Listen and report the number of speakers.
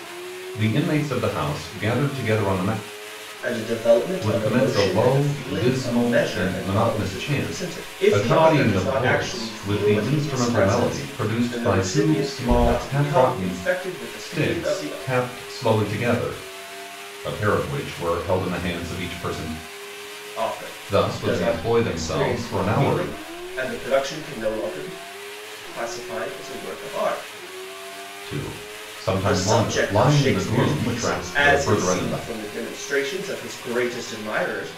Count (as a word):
two